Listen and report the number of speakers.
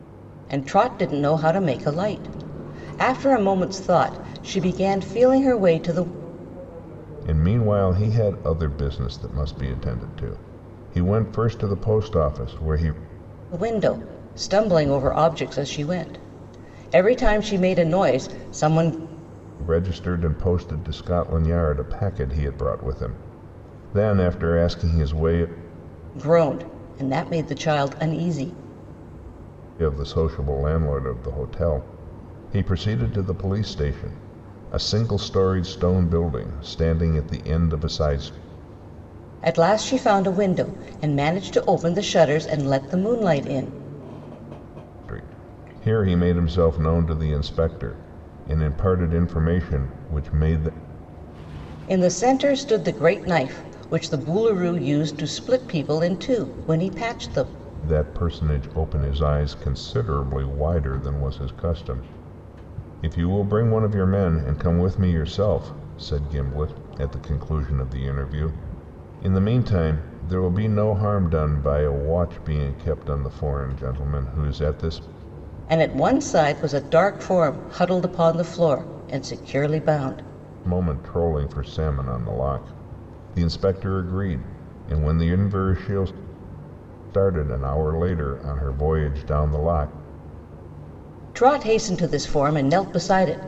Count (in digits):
2